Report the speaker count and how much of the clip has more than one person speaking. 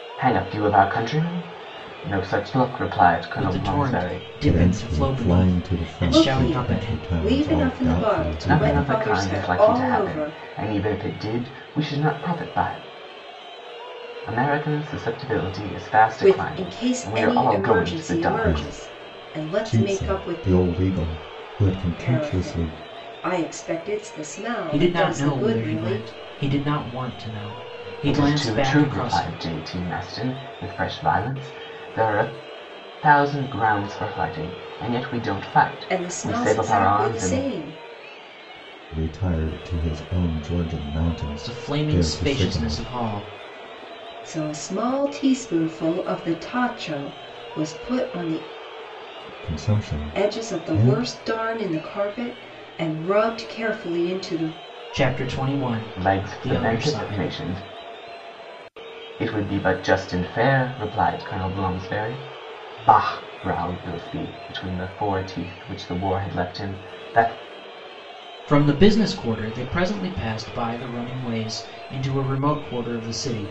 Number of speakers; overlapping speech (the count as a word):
four, about 27%